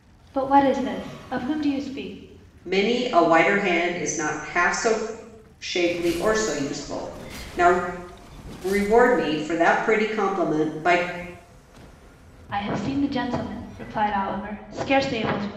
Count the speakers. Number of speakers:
2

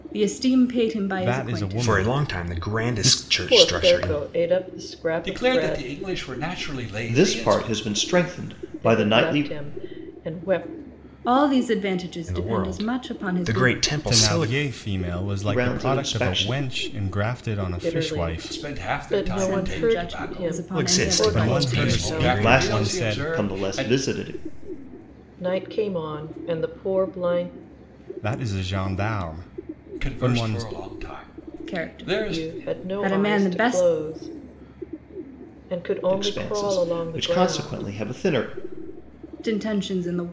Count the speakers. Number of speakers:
6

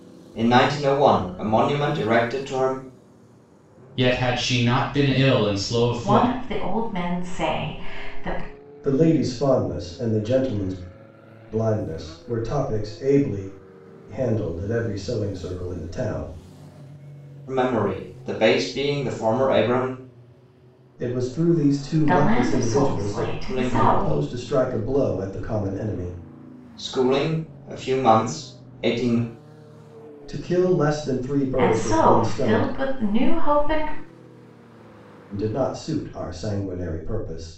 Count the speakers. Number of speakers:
4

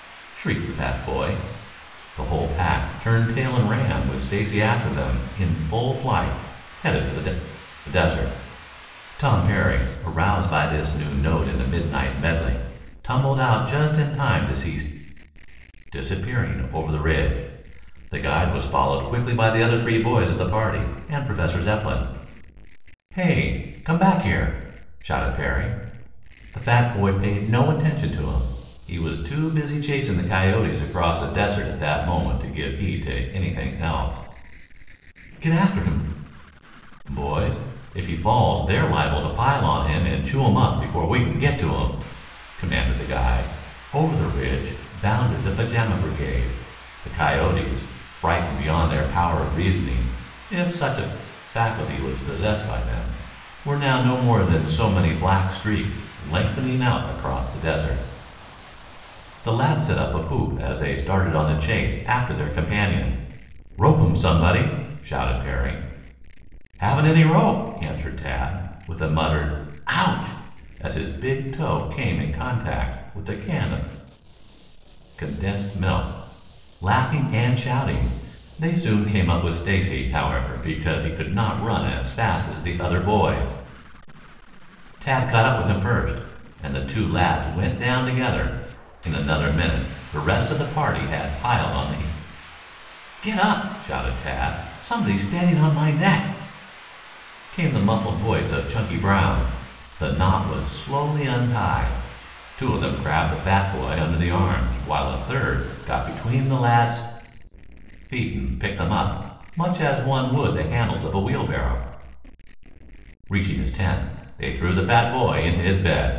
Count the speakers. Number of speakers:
1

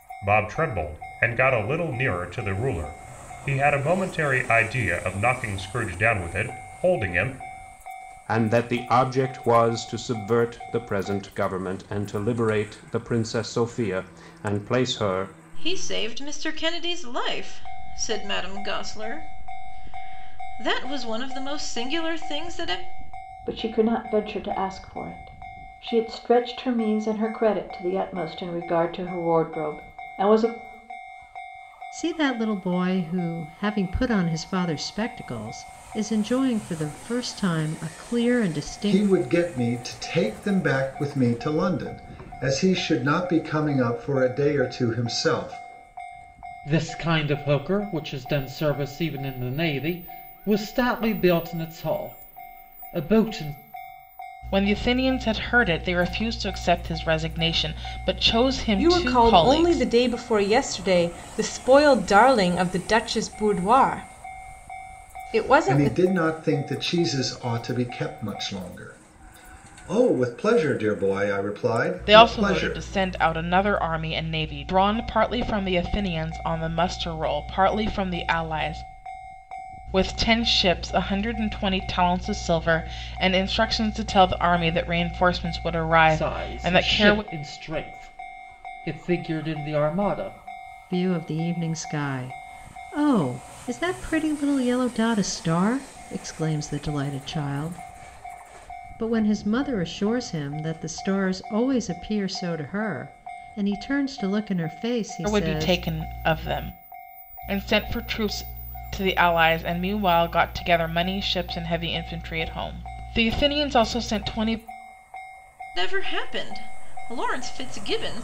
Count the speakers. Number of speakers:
9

